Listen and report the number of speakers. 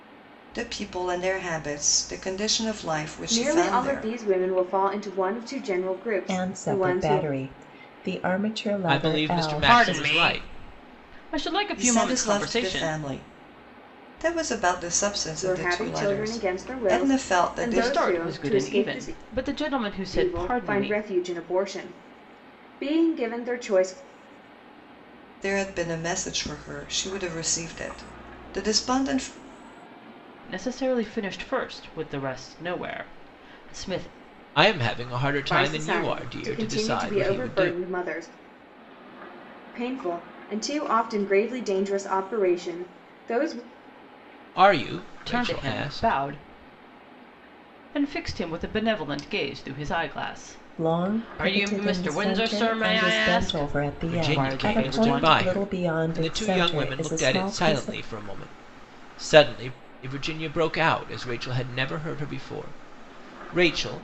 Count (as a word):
five